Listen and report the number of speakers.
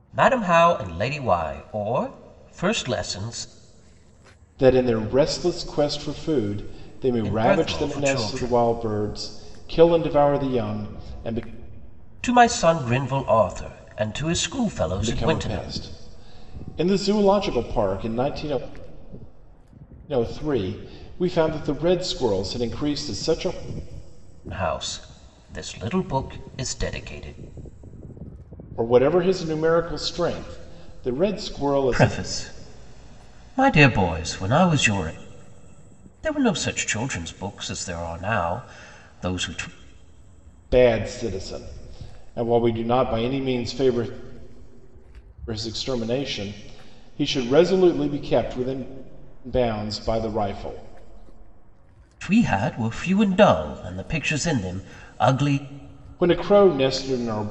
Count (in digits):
2